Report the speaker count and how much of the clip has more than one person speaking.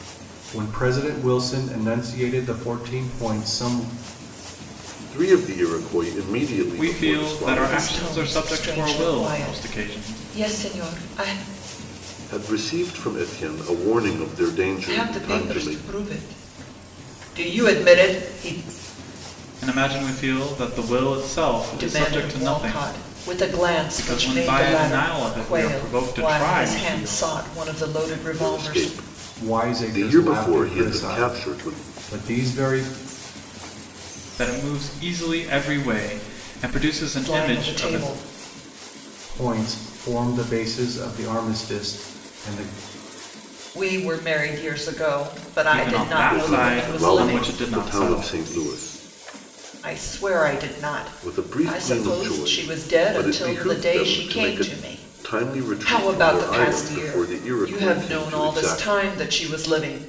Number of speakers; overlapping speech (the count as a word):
four, about 37%